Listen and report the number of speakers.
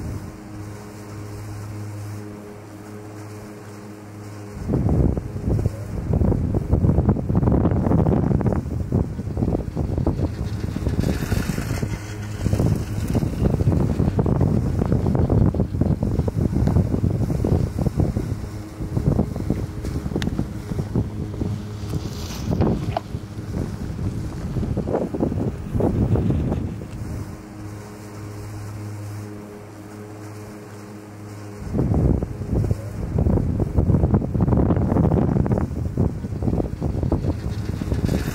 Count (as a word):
zero